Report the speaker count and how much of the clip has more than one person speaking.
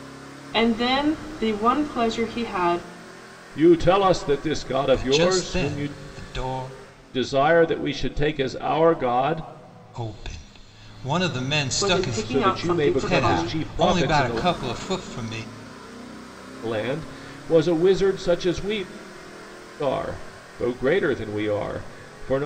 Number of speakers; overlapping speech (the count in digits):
3, about 17%